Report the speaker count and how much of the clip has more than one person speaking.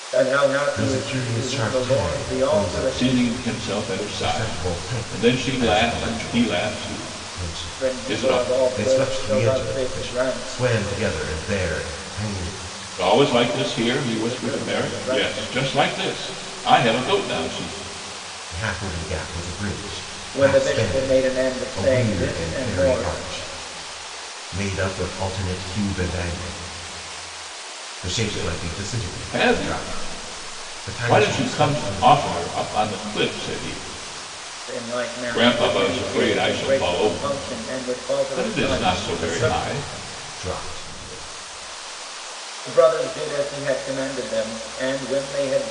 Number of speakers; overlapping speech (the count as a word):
three, about 42%